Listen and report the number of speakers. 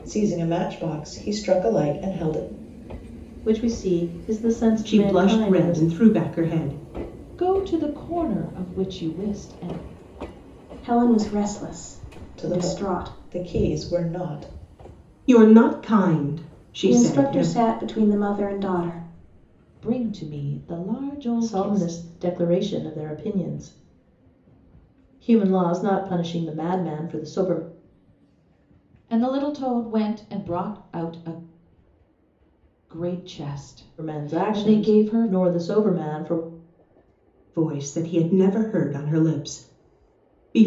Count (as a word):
five